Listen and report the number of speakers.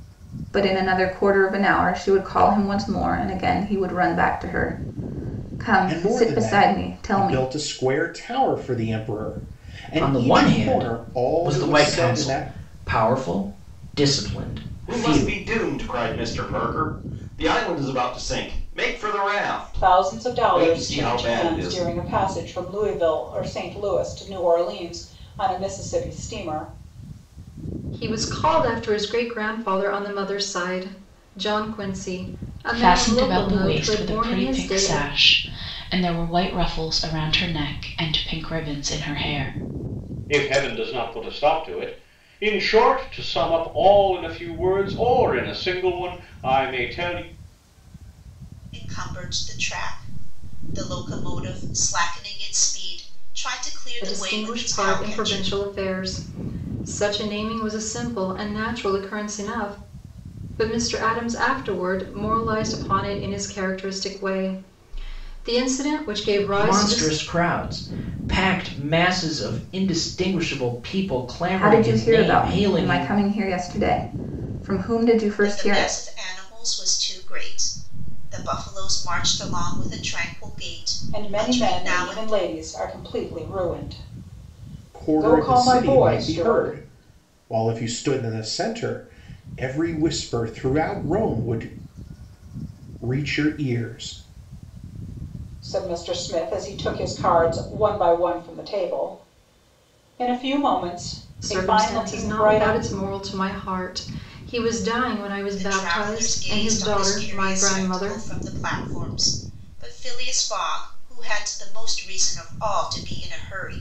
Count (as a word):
nine